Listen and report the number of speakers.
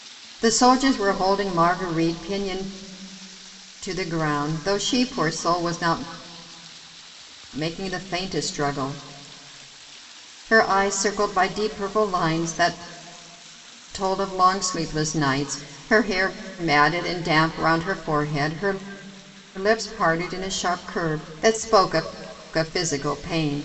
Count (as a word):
one